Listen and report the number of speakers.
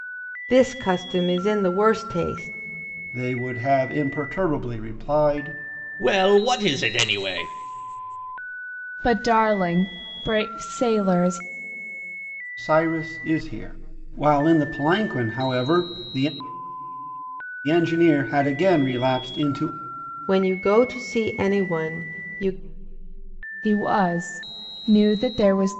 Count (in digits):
4